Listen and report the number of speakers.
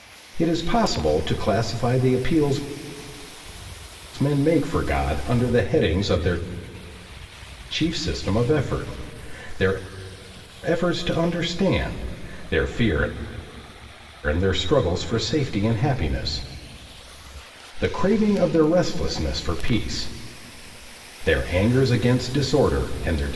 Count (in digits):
1